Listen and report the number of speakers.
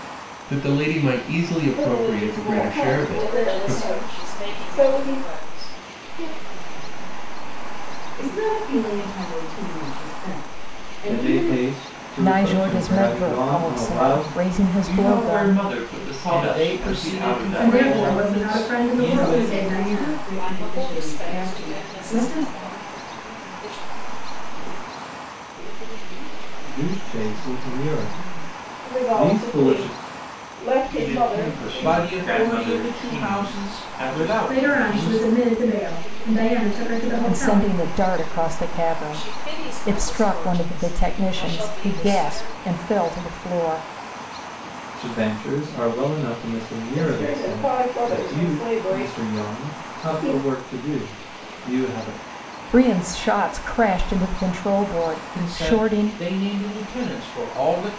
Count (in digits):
10